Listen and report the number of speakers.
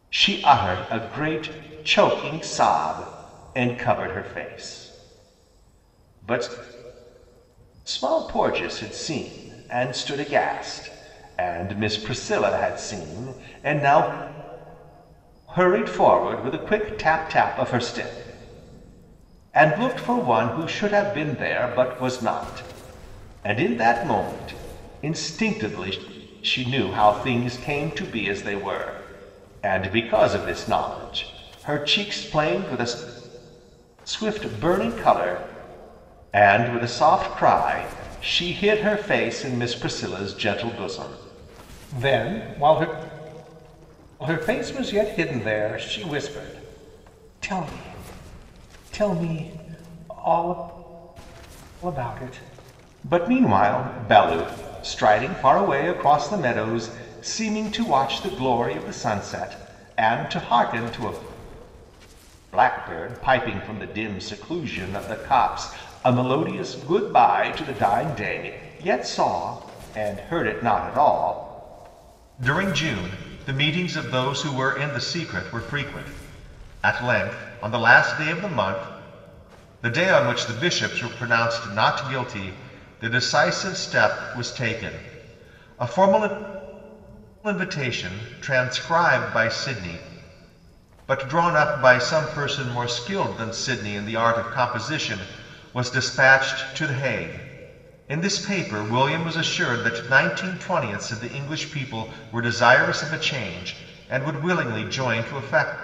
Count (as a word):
one